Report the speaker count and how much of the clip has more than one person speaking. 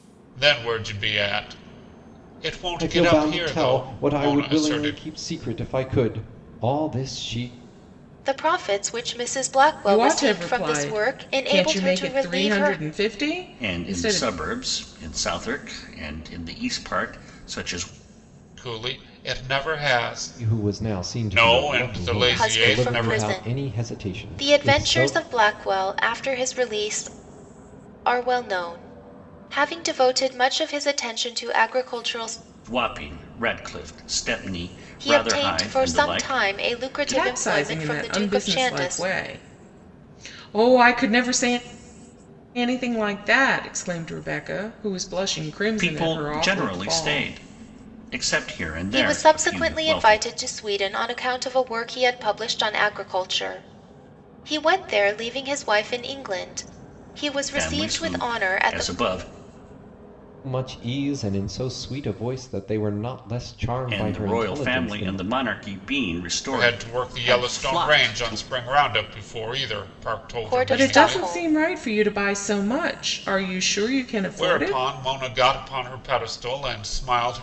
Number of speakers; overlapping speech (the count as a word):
five, about 31%